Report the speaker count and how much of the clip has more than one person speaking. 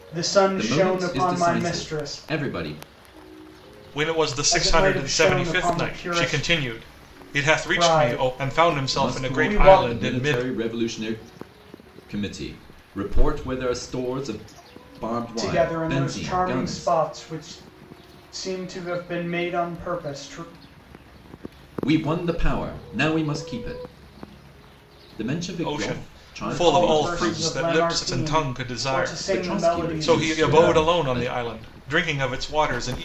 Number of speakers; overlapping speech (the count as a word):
three, about 41%